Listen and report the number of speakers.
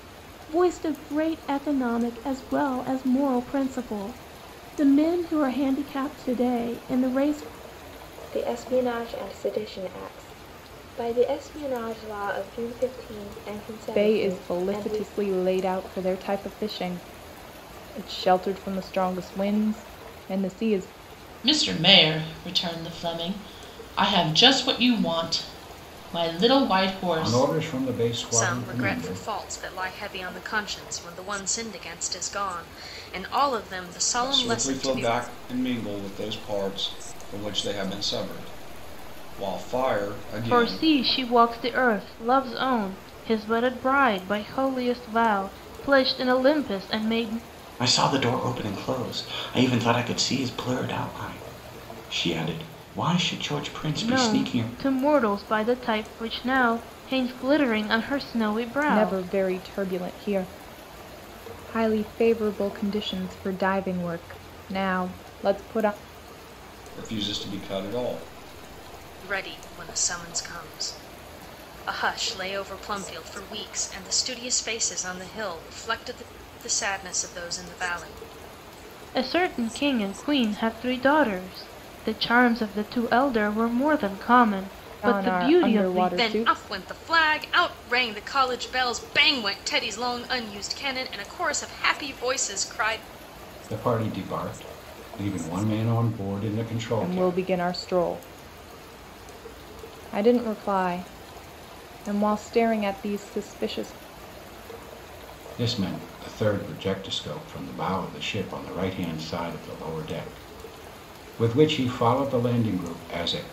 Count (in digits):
9